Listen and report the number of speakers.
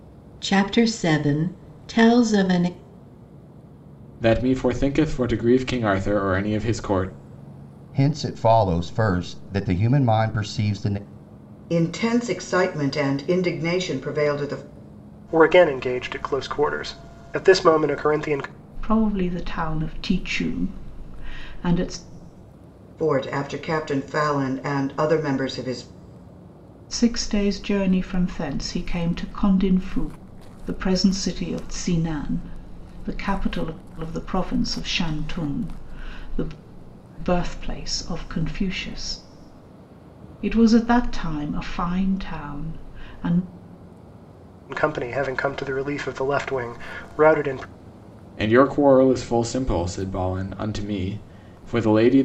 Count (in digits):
6